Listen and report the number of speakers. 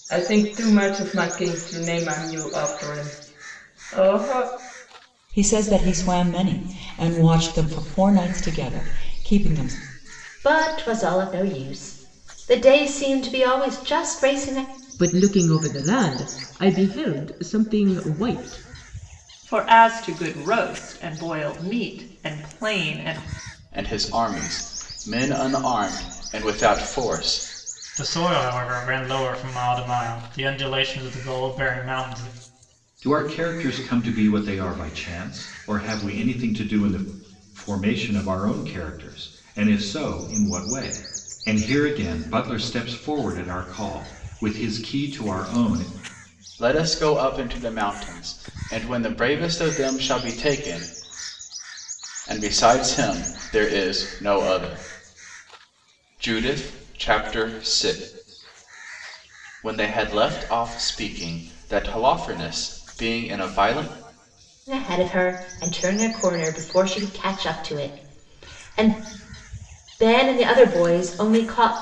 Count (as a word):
eight